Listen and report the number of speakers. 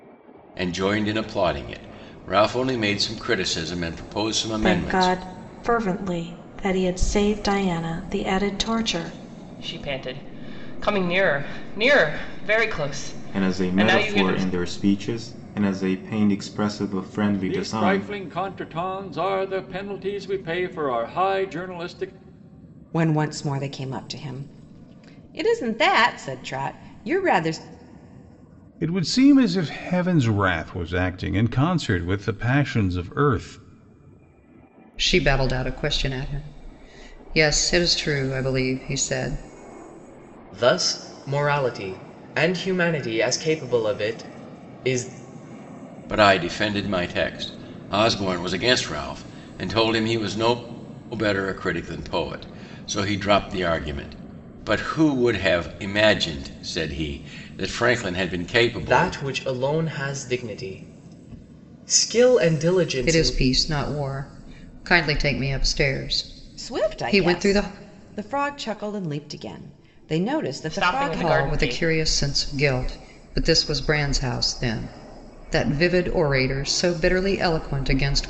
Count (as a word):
nine